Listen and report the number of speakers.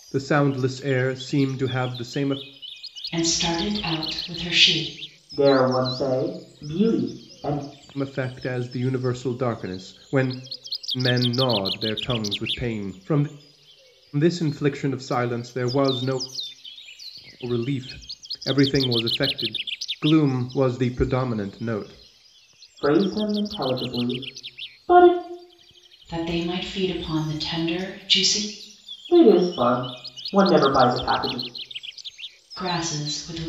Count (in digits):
3